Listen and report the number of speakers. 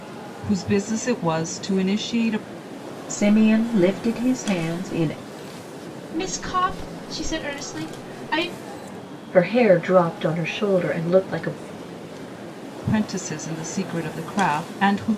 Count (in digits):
4